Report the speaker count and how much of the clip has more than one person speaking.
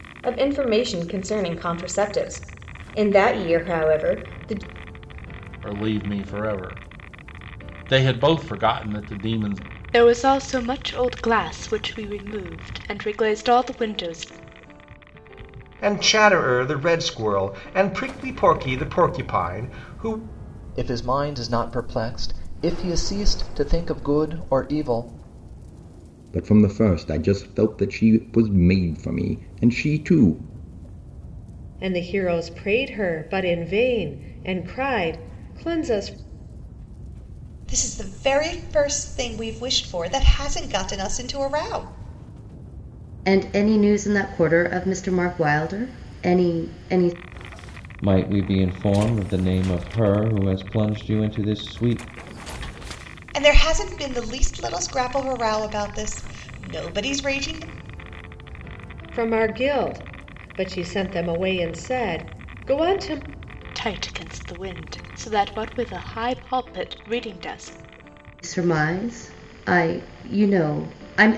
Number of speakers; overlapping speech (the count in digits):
10, no overlap